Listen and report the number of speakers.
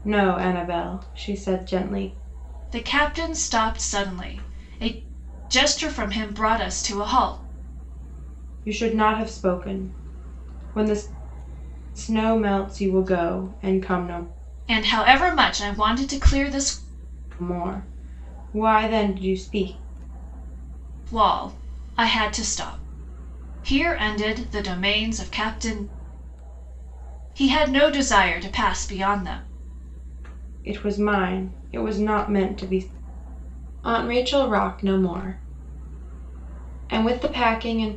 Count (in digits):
2